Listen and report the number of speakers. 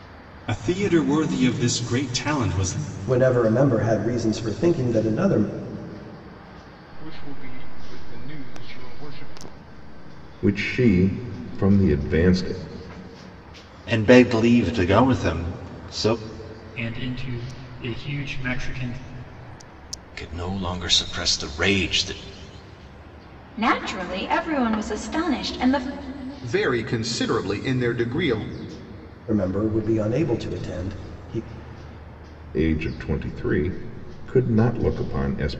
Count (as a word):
nine